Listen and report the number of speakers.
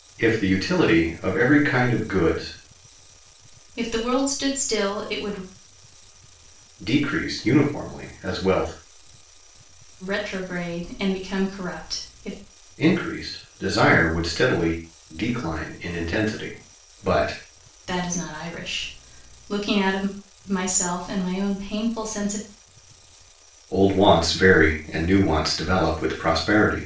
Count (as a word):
two